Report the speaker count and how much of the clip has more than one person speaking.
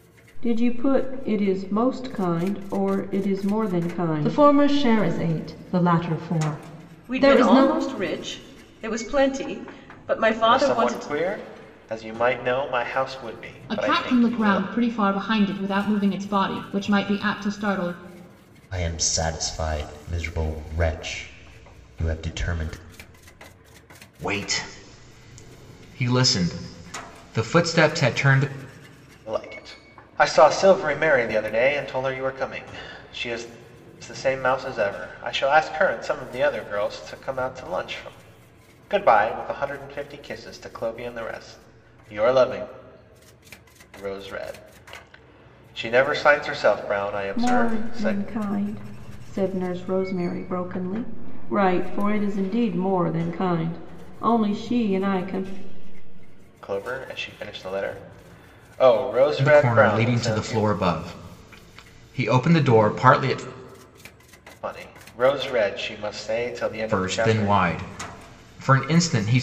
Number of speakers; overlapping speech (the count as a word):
seven, about 8%